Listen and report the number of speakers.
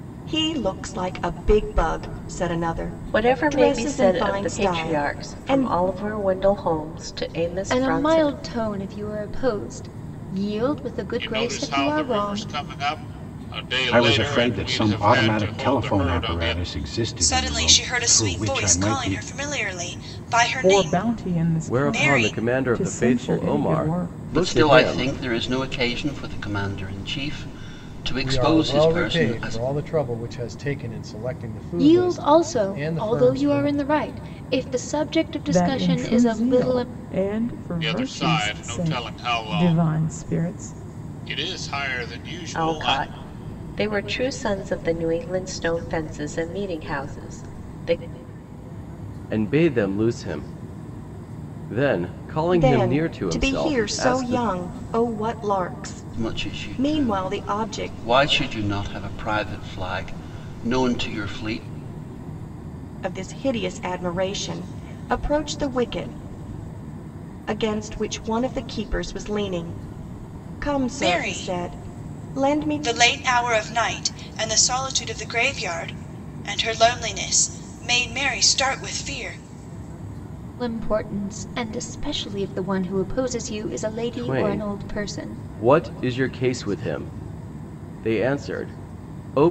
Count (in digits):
10